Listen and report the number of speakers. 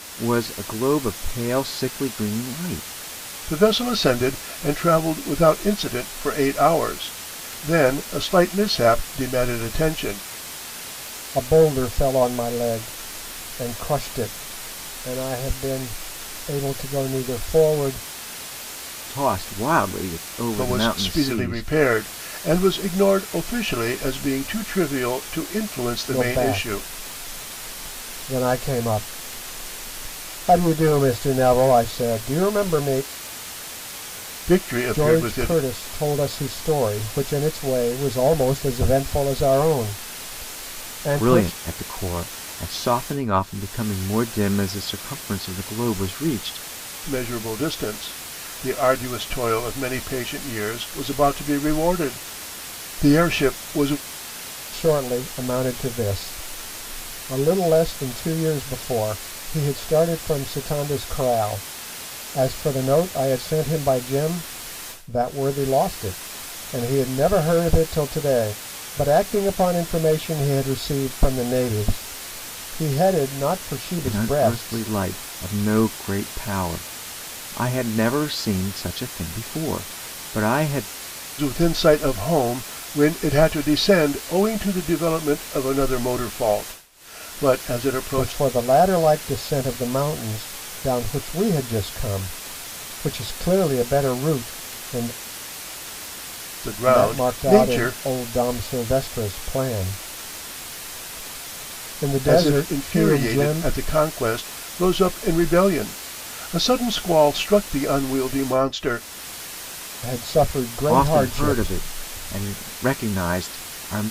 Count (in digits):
3